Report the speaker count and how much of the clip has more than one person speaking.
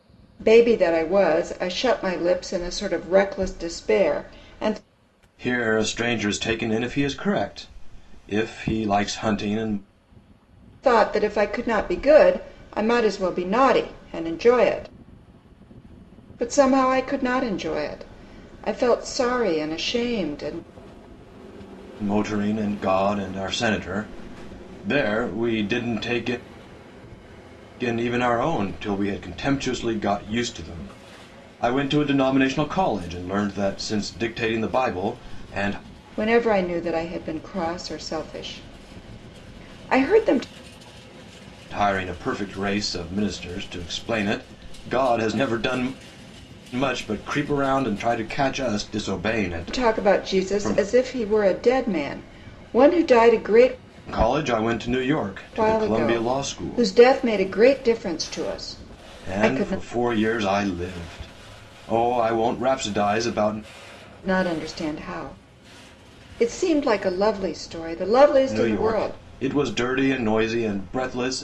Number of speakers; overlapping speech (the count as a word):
two, about 5%